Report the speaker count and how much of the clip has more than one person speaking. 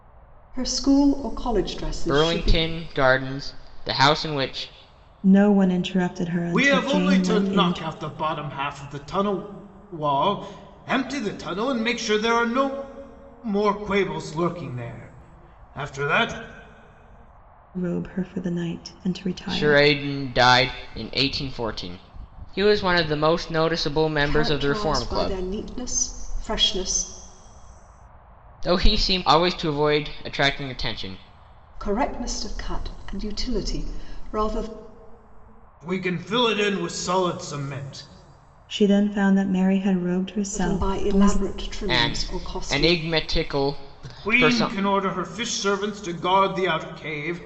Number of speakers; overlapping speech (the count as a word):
four, about 14%